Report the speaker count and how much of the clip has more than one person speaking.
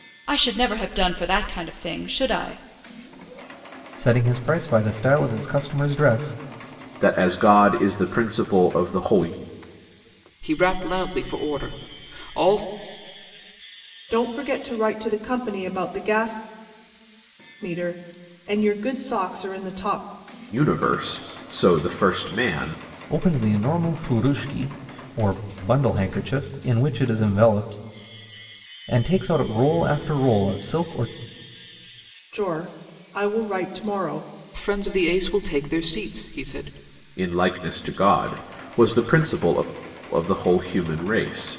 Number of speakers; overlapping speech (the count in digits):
5, no overlap